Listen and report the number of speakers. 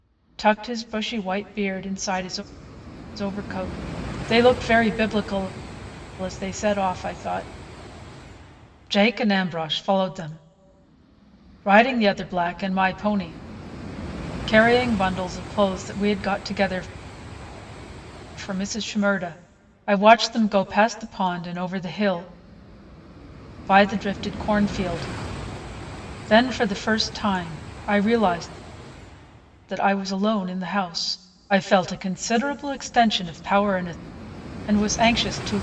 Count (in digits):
1